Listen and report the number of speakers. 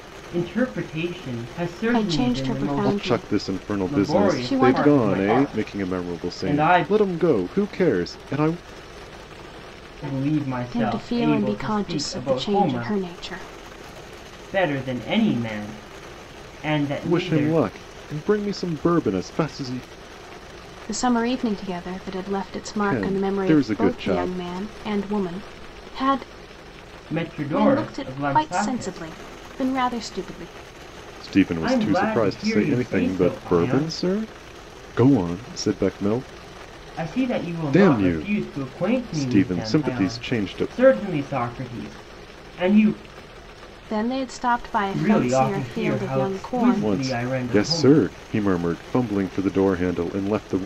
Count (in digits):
3